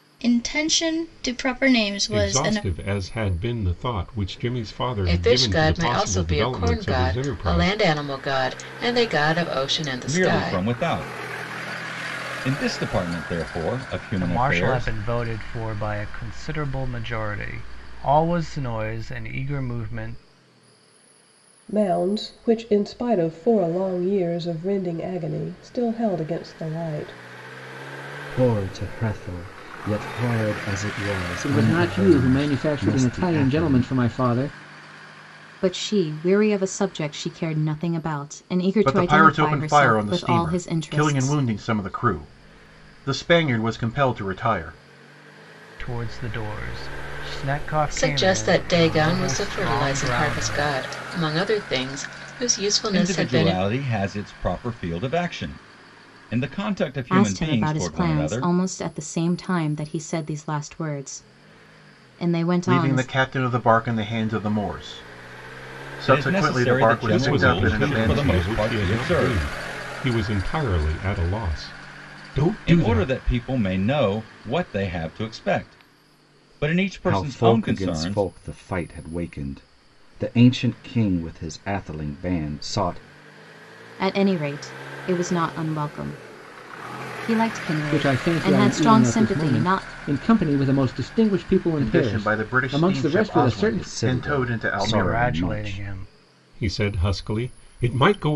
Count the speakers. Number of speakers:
10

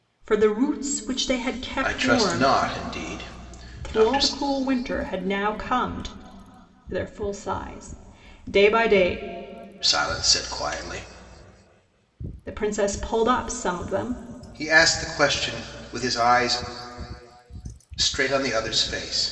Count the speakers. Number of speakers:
2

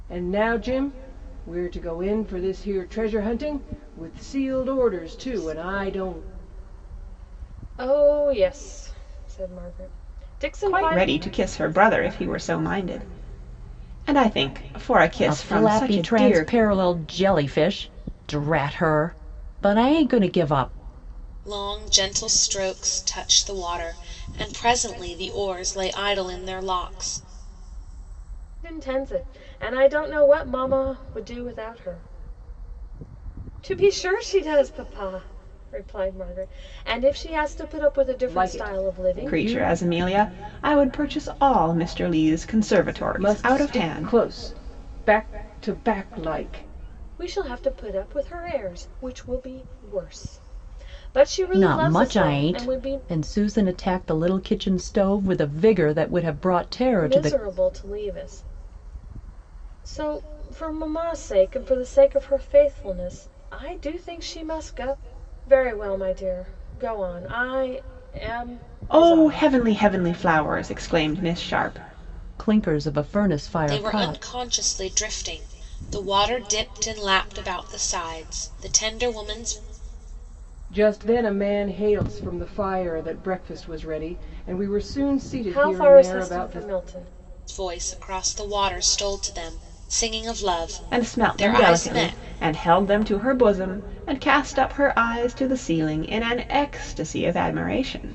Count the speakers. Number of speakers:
5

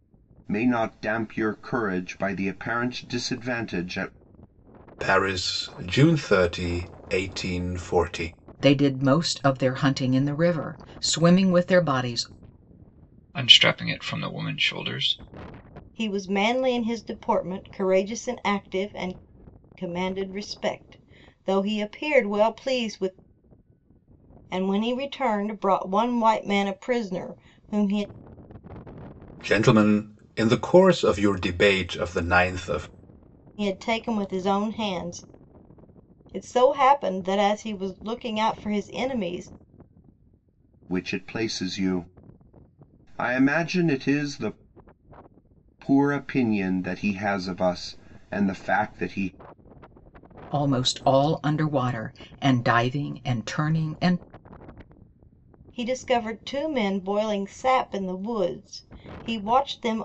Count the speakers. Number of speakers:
5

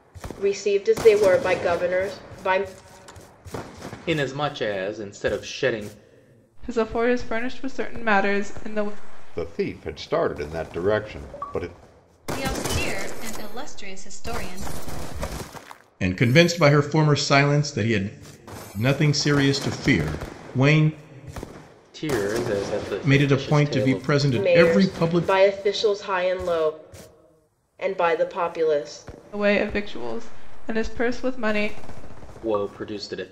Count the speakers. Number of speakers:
6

